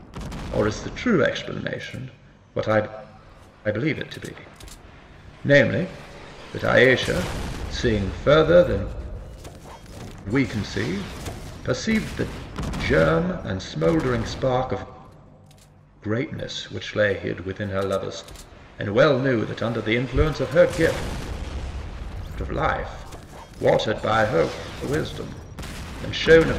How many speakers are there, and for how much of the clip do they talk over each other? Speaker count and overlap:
1, no overlap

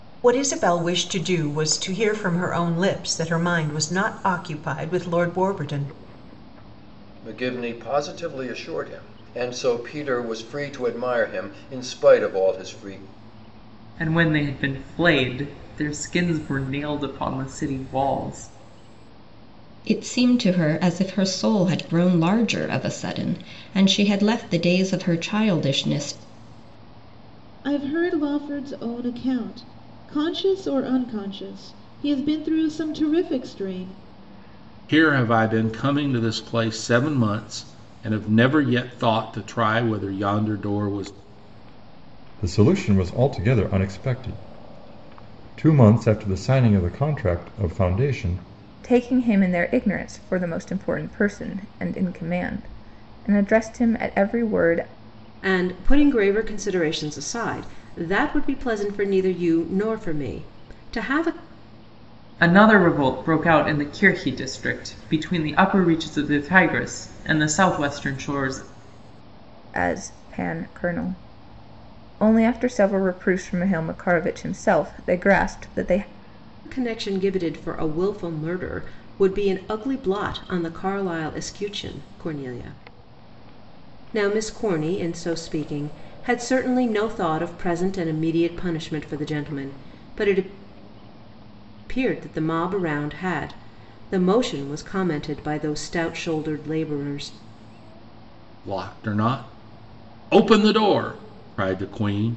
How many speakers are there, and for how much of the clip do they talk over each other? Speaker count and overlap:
9, no overlap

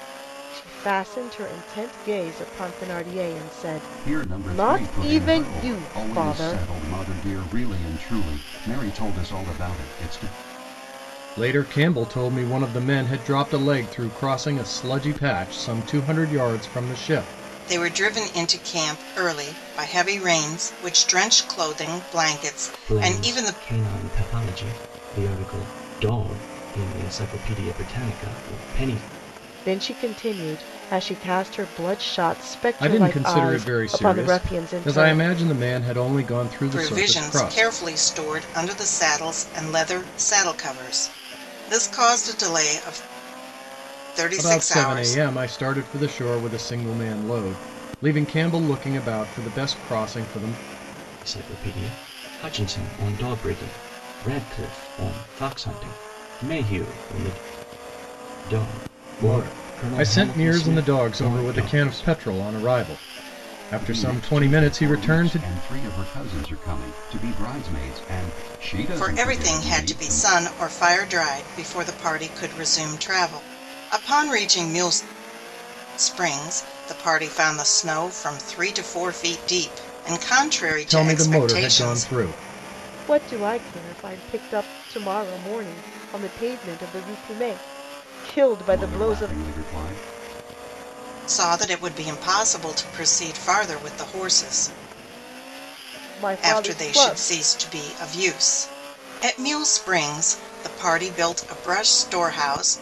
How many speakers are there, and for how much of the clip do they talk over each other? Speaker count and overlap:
5, about 16%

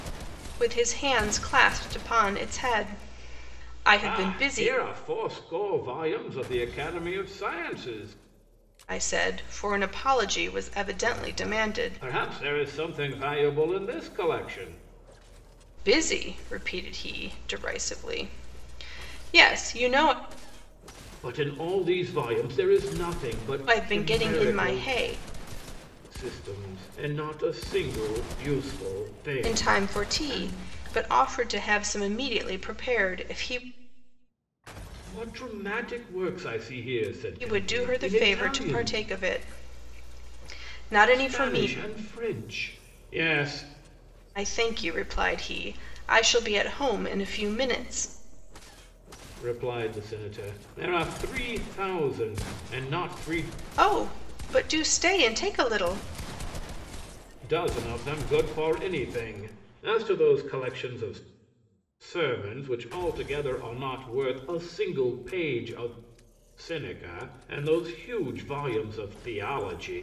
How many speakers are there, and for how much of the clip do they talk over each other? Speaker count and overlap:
2, about 9%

